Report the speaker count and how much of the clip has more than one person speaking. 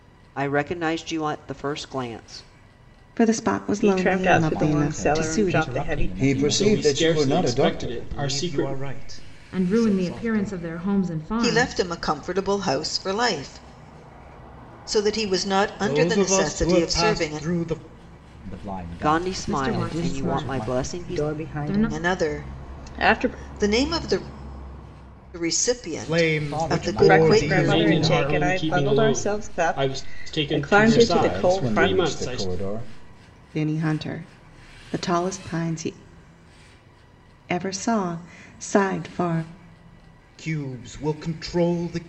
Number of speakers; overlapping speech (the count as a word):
nine, about 45%